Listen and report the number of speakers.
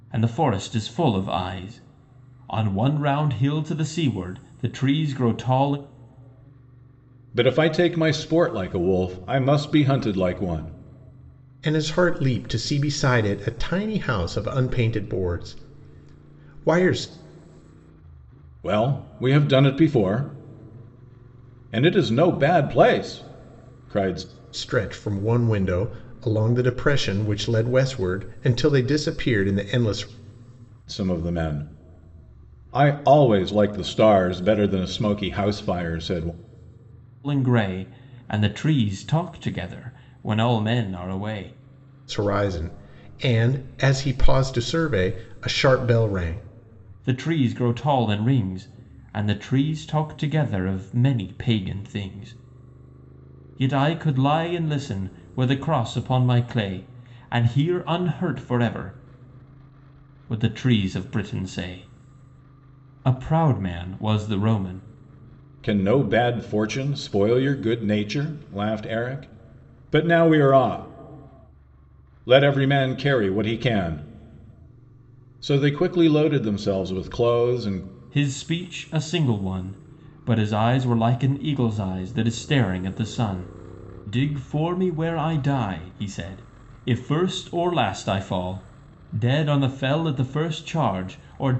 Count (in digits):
3